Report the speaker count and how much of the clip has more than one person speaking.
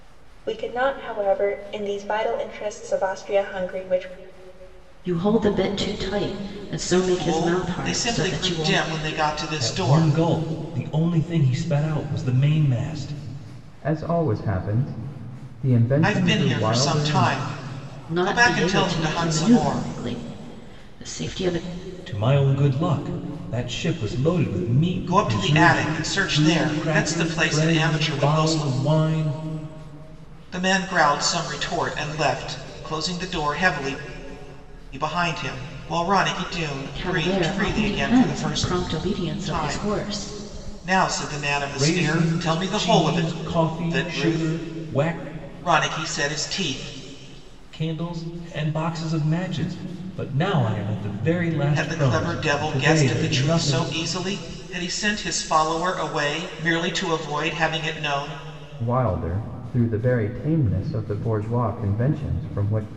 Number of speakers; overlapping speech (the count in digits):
5, about 27%